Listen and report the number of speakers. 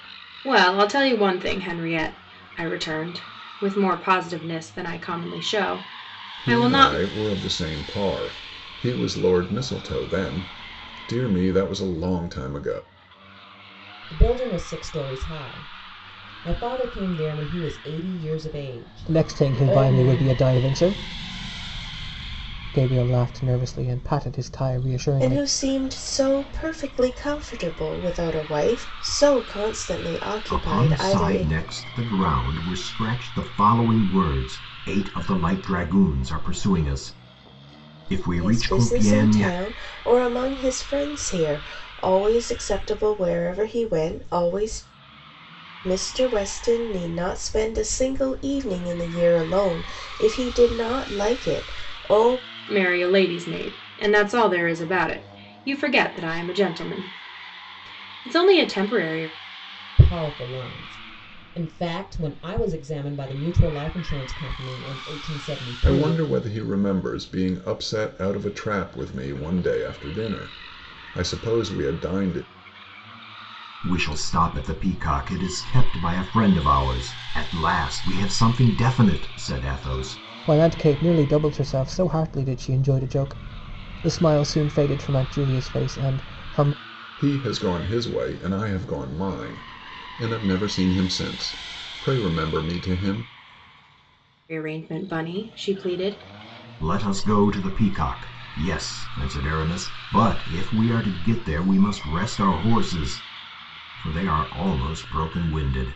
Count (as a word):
six